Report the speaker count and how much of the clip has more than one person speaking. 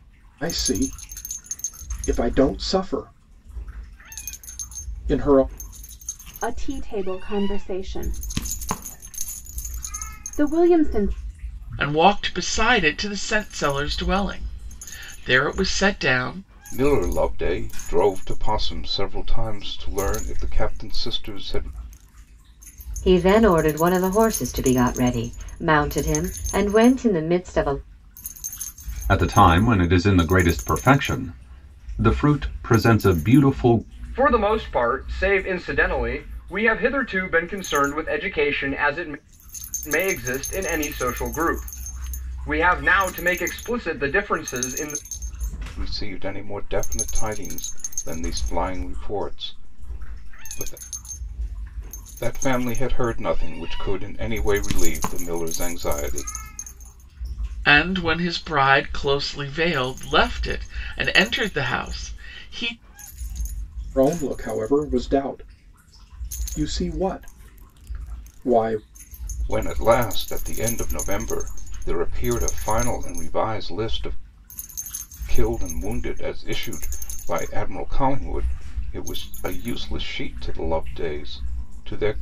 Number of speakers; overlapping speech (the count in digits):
7, no overlap